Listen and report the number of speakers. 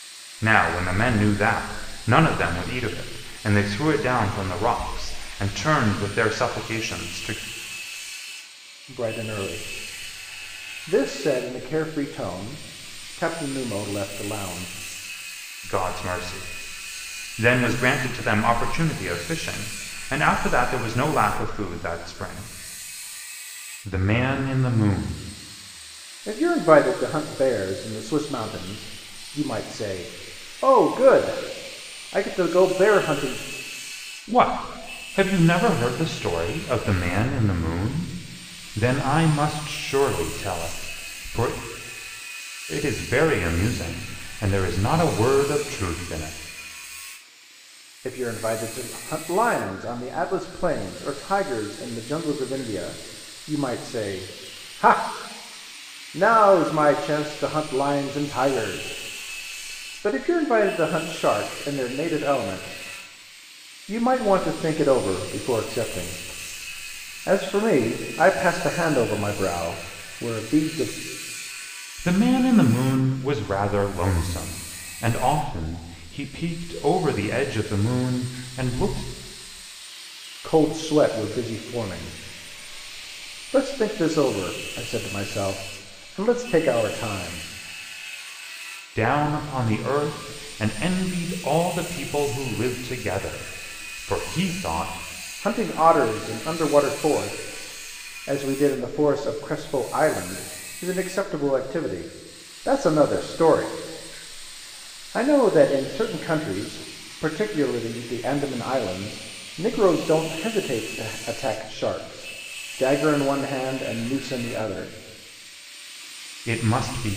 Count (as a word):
two